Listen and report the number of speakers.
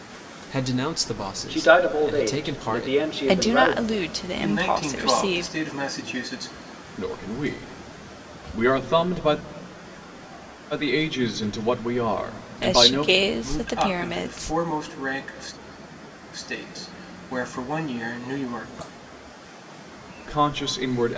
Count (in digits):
5